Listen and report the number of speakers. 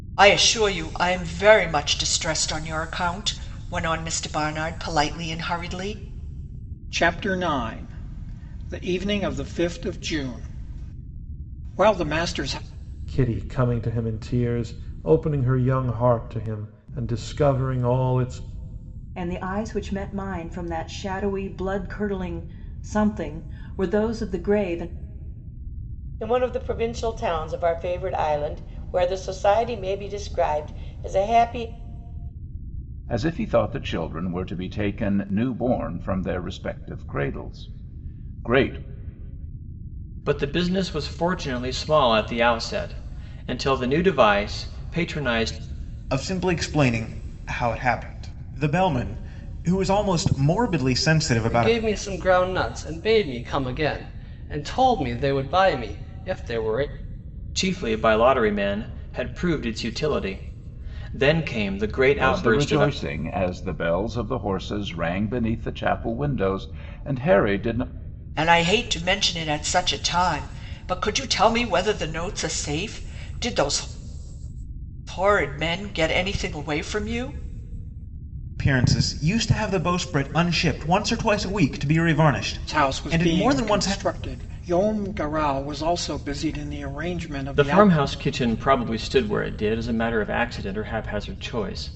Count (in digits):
9